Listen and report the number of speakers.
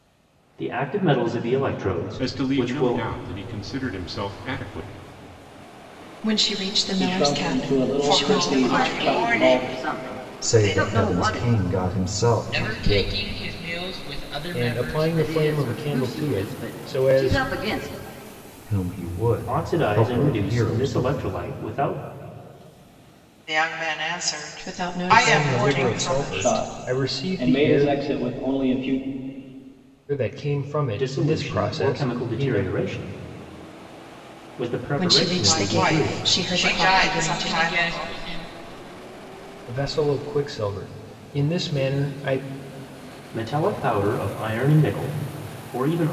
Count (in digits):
9